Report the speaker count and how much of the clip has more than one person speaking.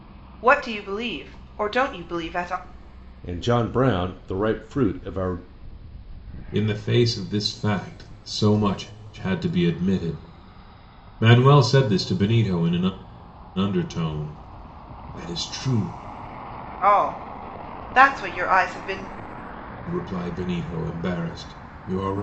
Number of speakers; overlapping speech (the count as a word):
three, no overlap